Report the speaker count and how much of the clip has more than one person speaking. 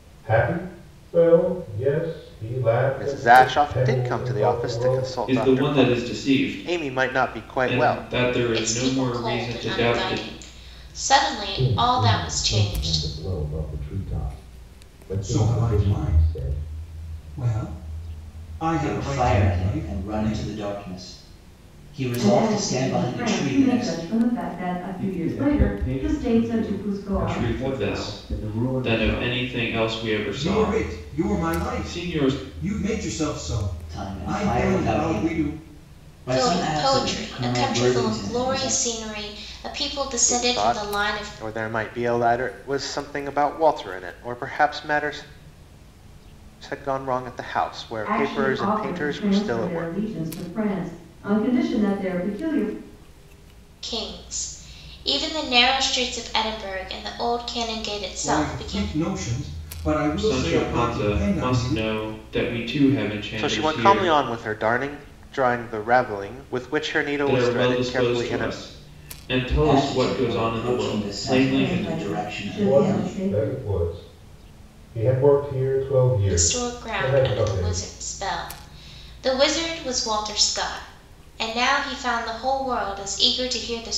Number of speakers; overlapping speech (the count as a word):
nine, about 44%